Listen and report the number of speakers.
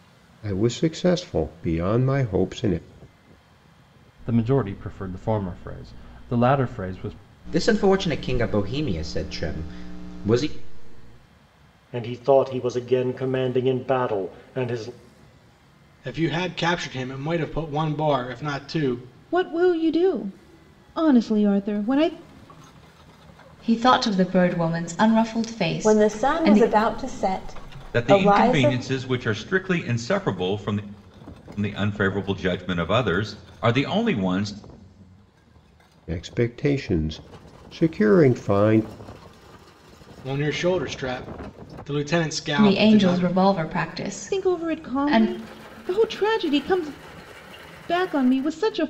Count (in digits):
9